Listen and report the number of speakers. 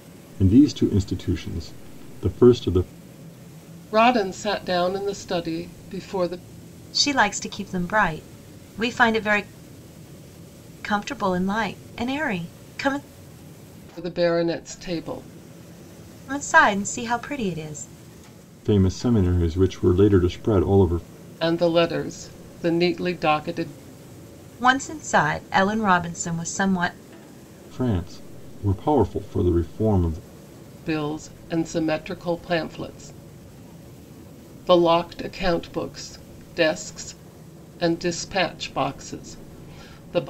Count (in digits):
3